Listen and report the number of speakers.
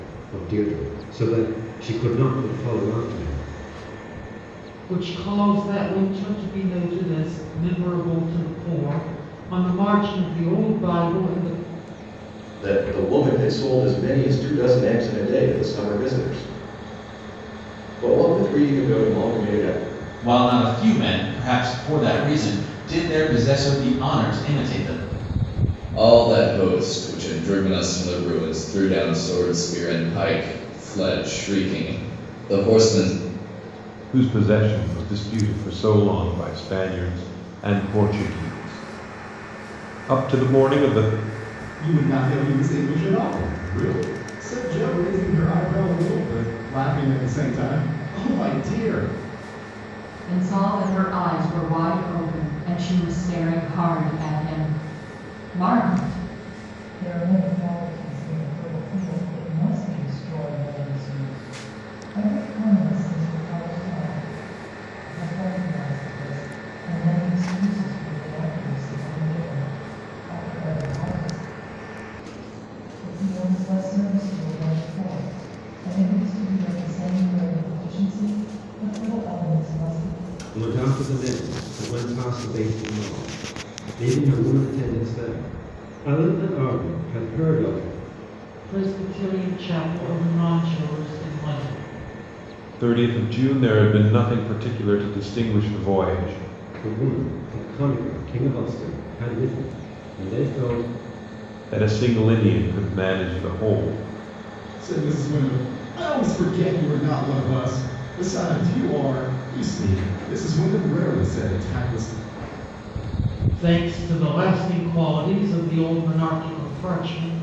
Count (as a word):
nine